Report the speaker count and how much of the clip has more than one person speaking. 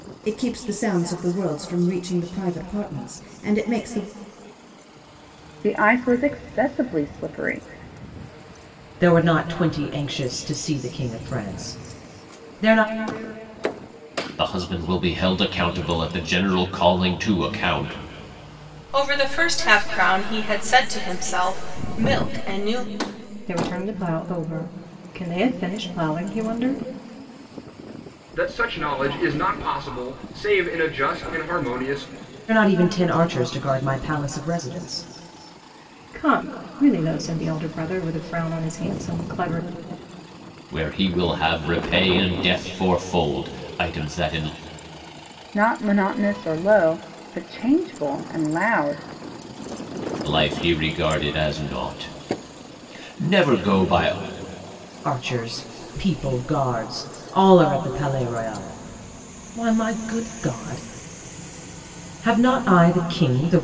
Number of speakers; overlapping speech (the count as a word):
seven, no overlap